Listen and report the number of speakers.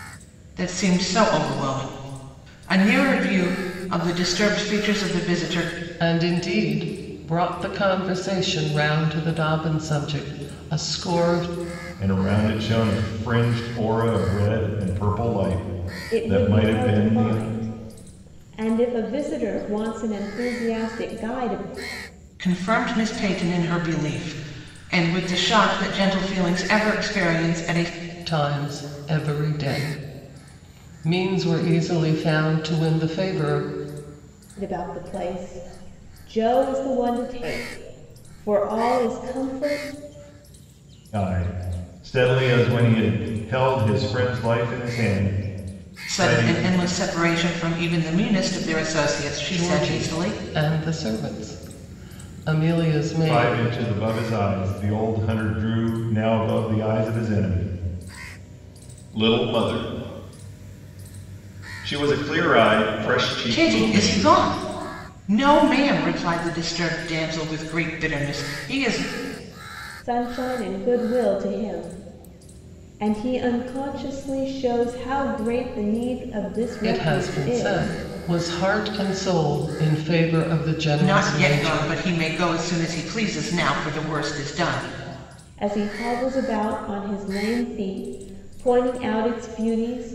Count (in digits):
4